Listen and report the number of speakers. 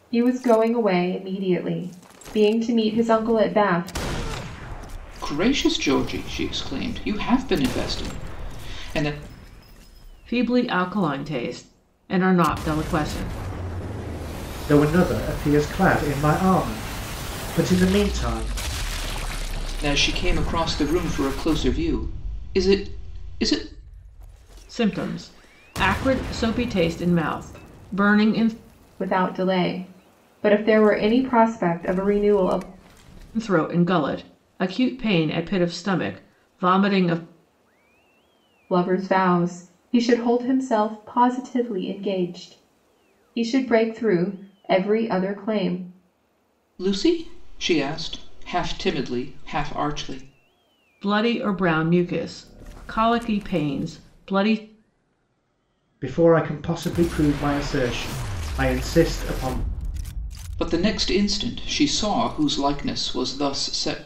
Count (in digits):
4